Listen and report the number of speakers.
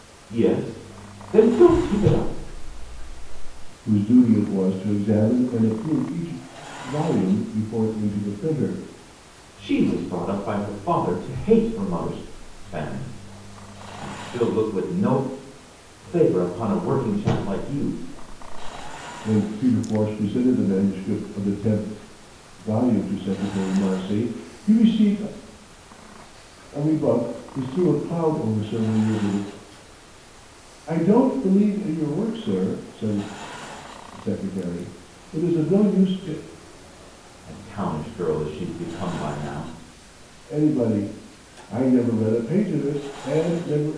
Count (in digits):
2